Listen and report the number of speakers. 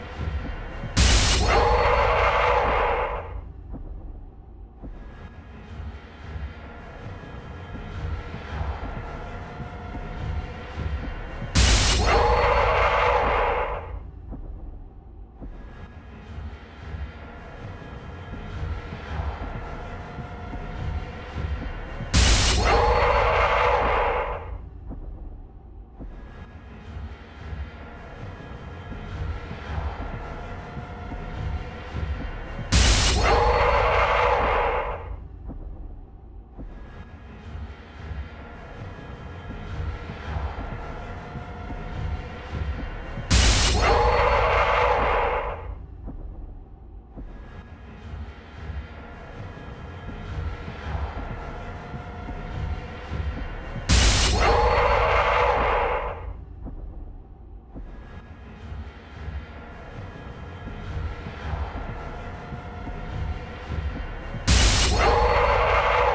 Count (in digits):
0